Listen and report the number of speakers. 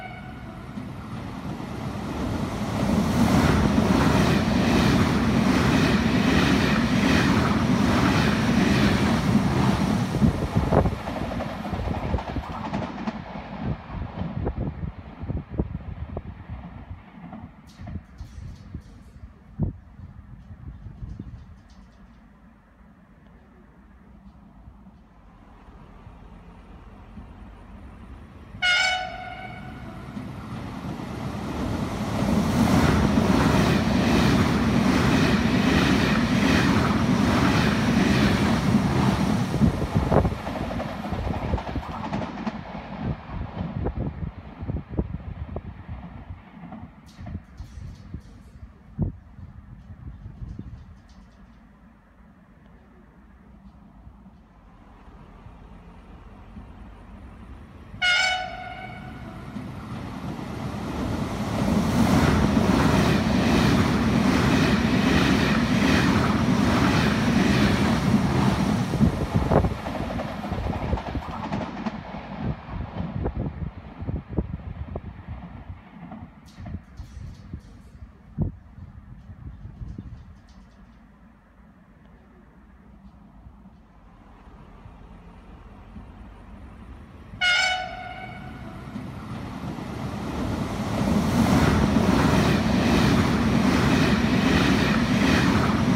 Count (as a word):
zero